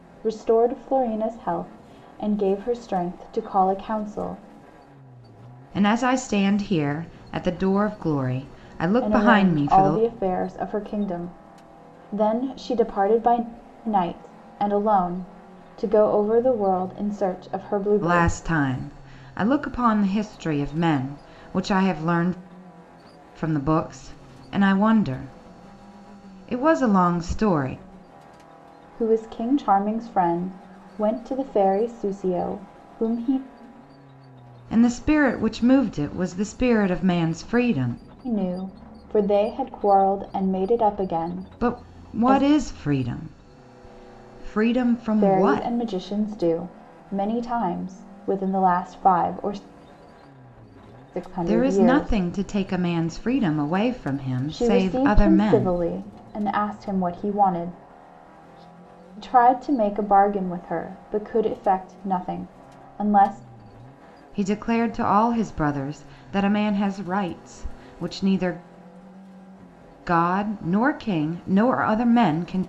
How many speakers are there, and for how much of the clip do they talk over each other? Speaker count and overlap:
two, about 7%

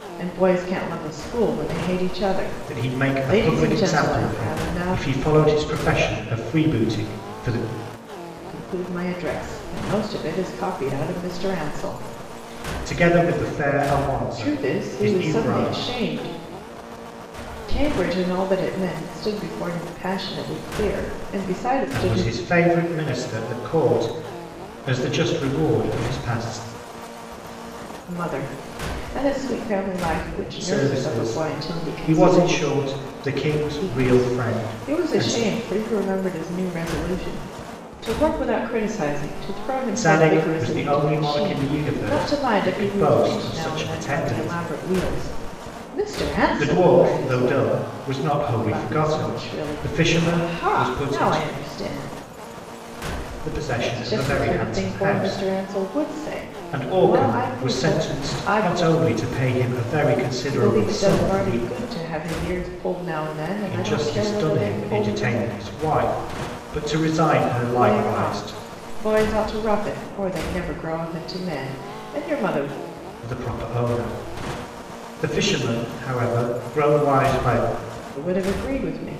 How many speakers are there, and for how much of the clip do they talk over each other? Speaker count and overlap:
two, about 32%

